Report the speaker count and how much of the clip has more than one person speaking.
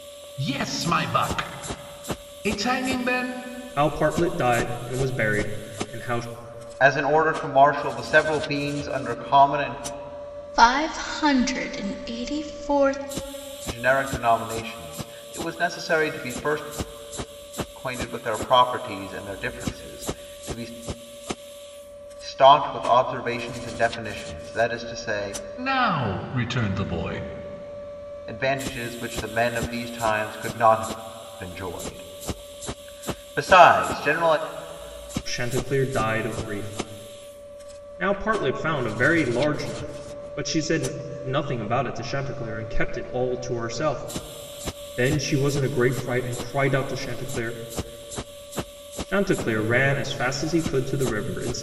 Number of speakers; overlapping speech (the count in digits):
4, no overlap